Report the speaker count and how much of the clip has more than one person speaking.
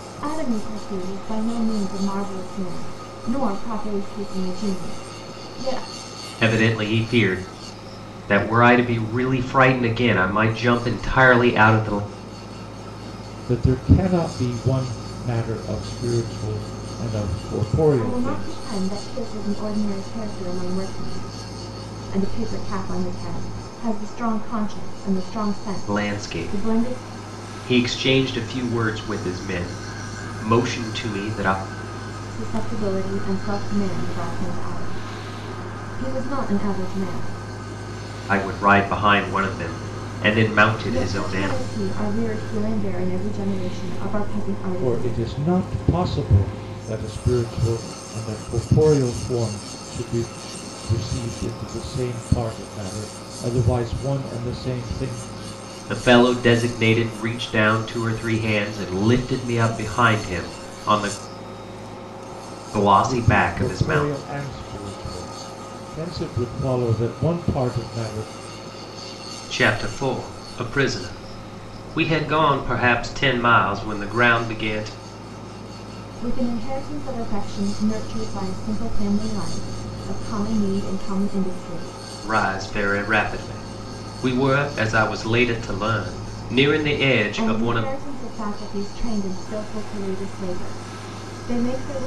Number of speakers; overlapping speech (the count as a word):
three, about 6%